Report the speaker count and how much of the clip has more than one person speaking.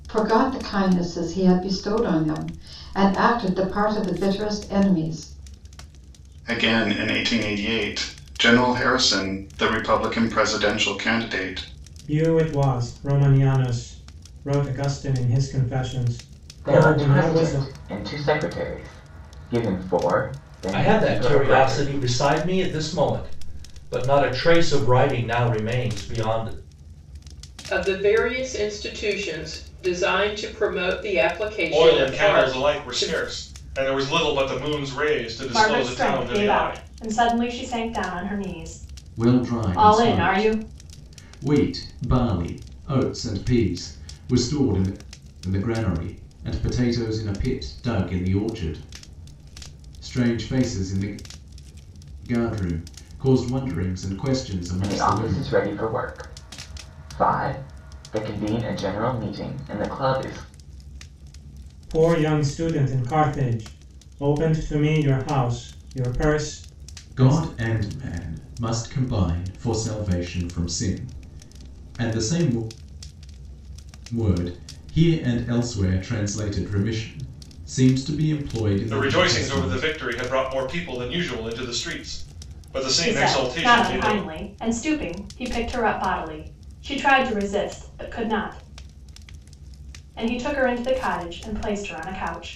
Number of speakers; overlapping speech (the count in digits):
9, about 11%